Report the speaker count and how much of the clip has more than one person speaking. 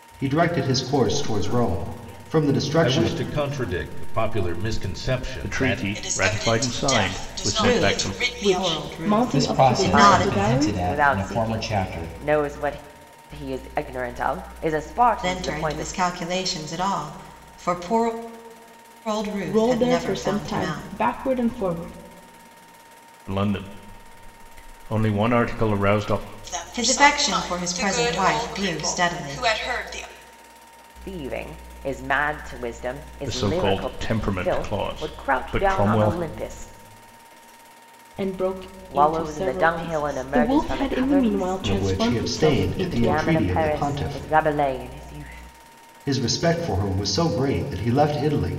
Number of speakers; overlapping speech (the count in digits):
9, about 47%